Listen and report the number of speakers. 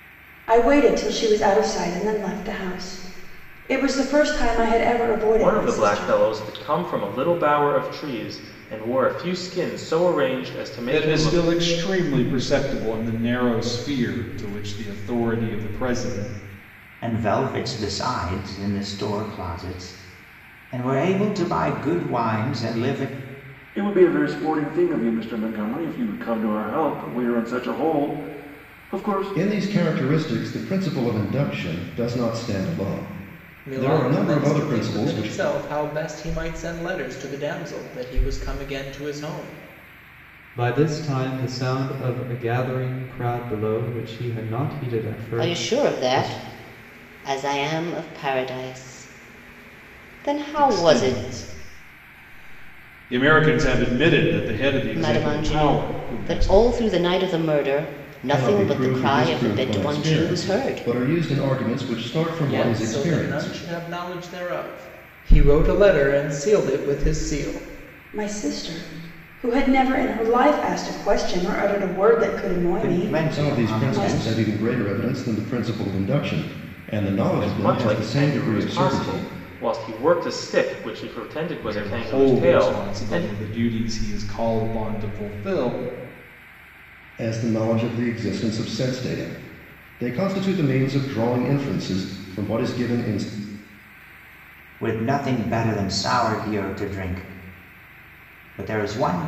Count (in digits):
9